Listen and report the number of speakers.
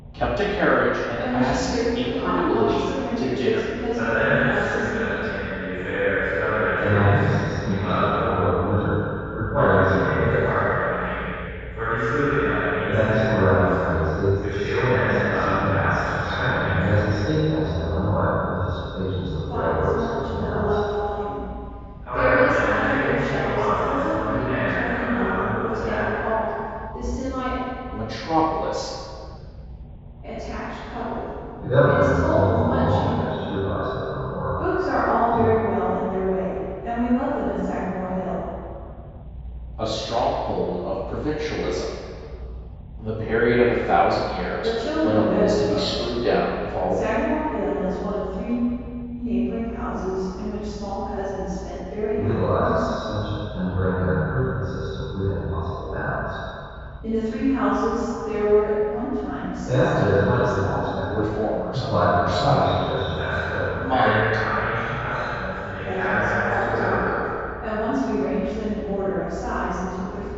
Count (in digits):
4